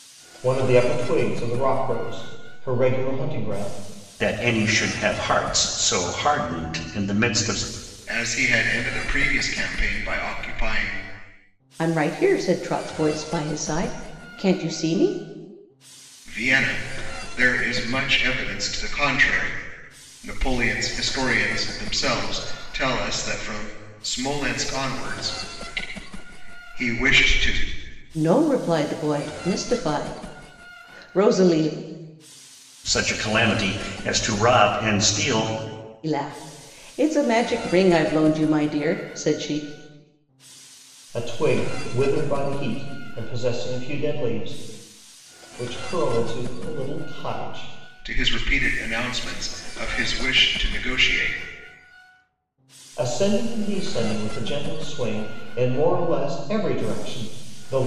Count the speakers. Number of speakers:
four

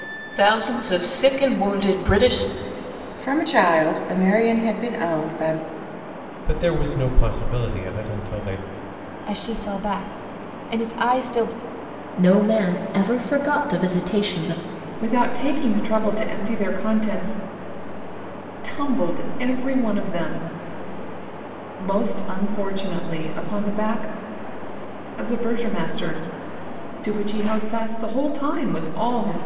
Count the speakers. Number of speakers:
six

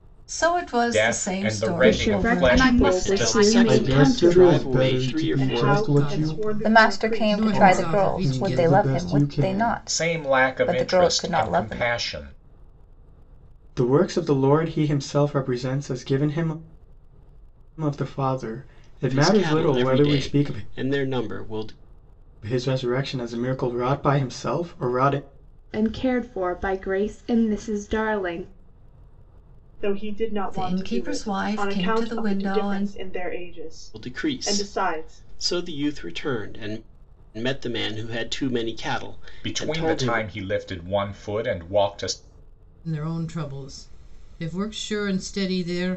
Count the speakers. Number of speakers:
nine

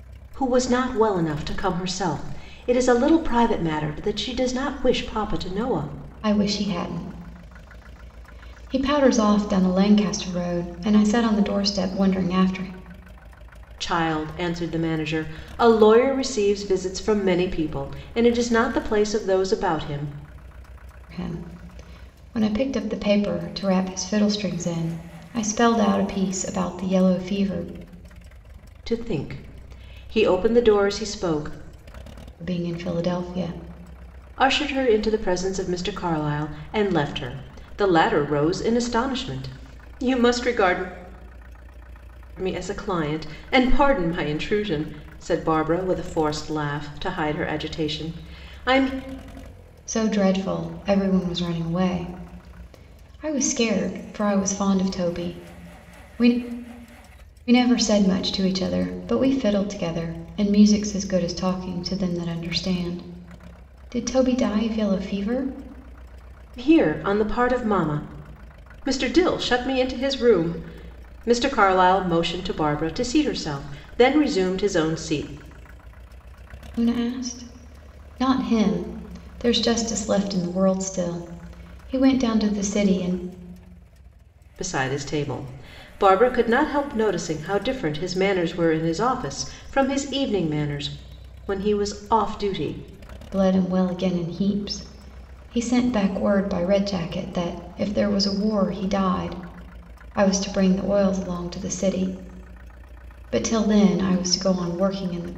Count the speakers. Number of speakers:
two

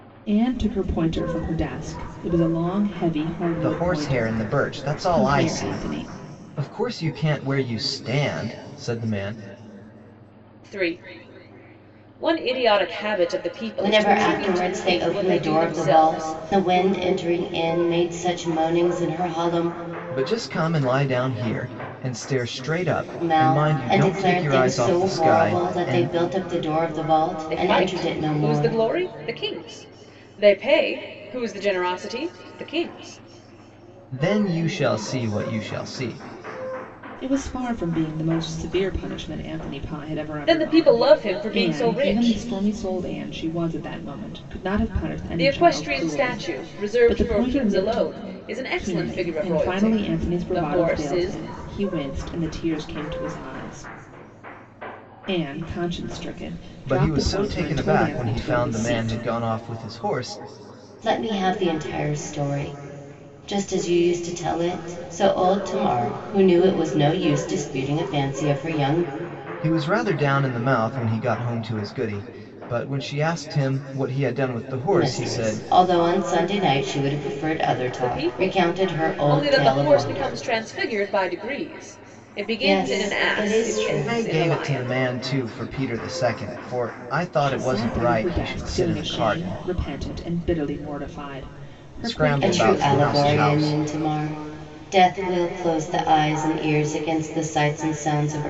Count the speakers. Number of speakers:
four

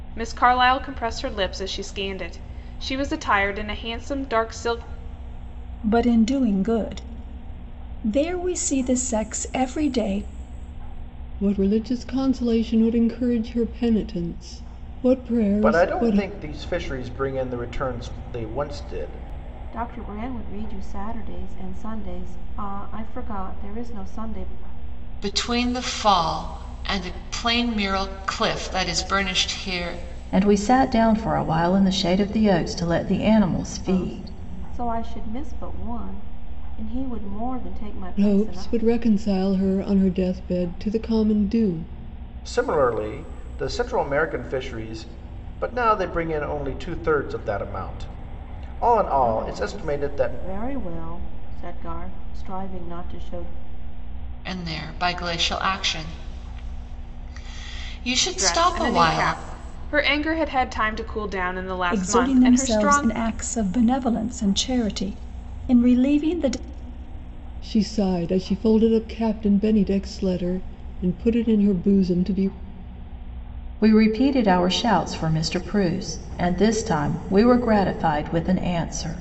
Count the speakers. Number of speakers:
seven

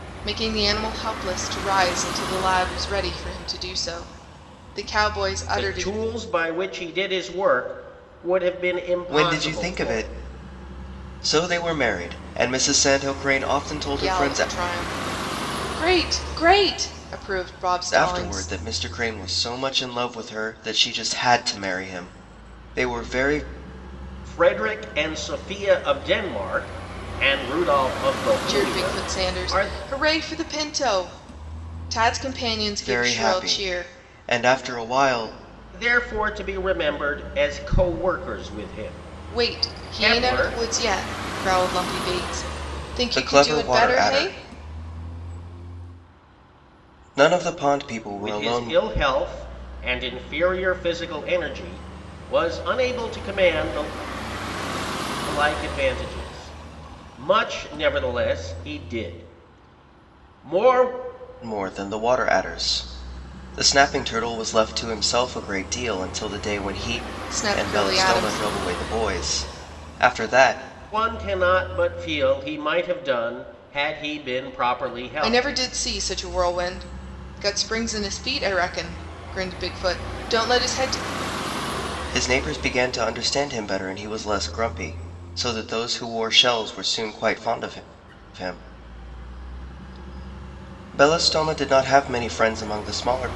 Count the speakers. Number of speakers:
three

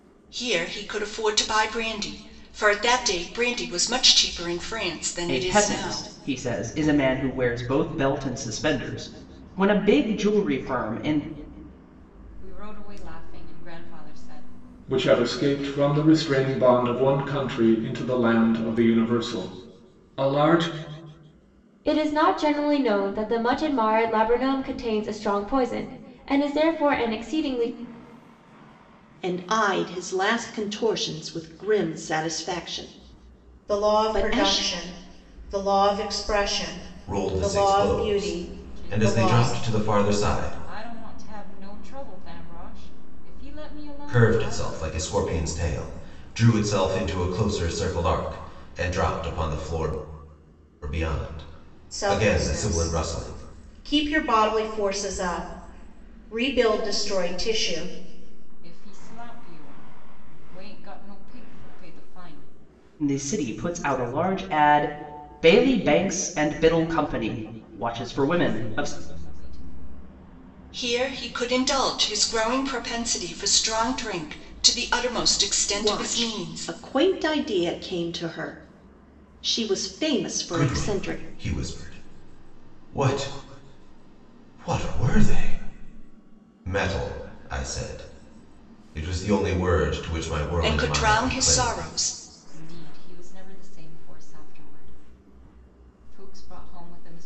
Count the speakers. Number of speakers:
eight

